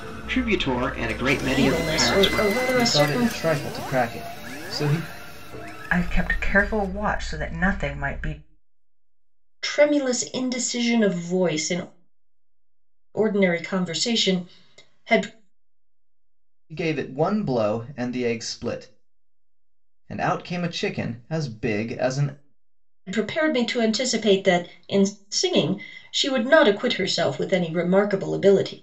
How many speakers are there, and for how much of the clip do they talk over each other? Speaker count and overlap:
four, about 6%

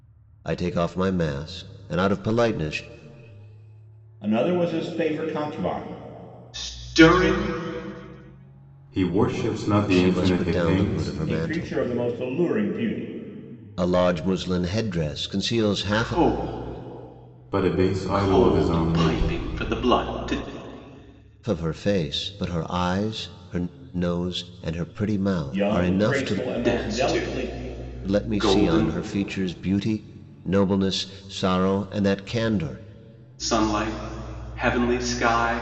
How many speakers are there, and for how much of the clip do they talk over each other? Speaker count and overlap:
four, about 18%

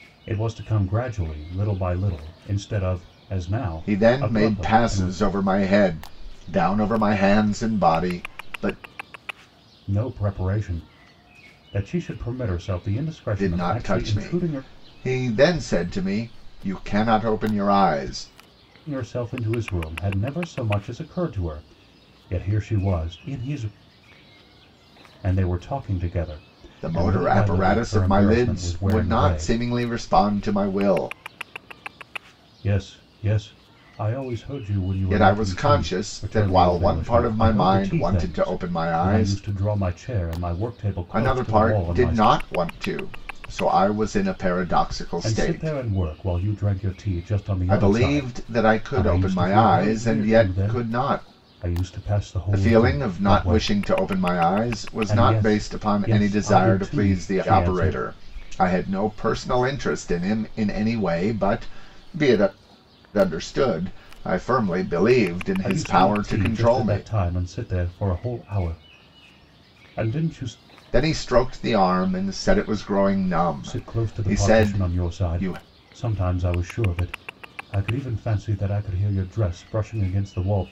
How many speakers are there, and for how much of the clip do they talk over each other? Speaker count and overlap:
two, about 28%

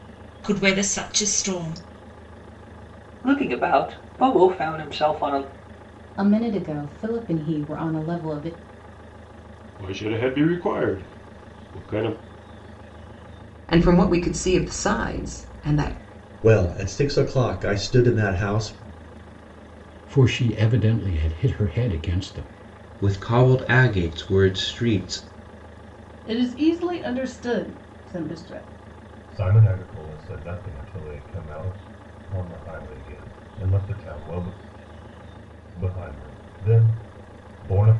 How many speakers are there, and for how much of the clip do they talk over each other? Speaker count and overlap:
ten, no overlap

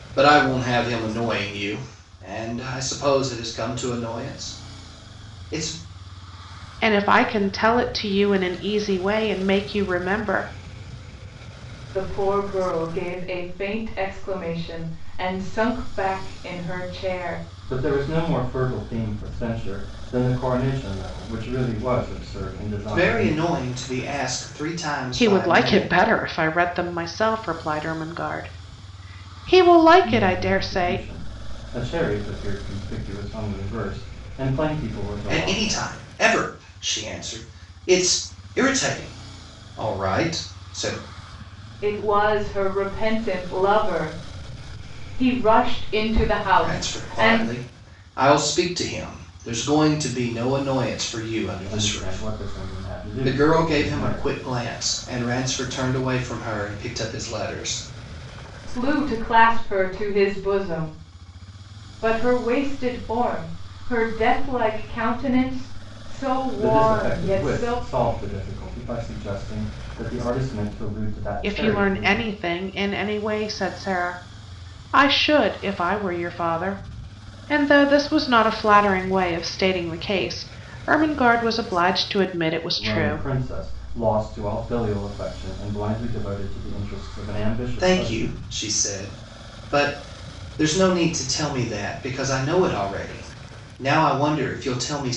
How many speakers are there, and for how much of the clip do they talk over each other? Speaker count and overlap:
four, about 9%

